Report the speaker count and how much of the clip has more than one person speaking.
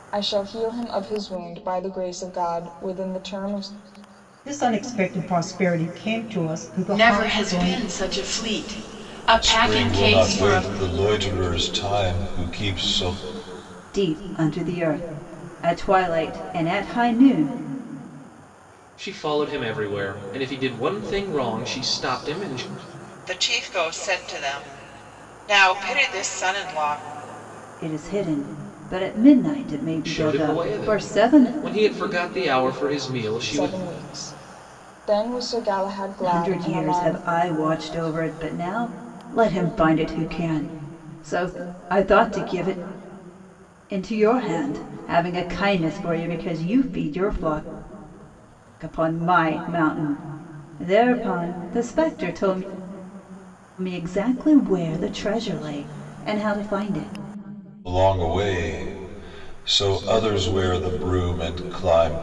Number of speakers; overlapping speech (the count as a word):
seven, about 8%